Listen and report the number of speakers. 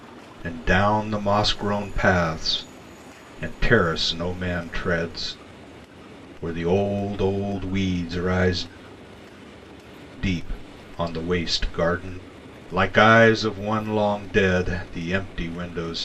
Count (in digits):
1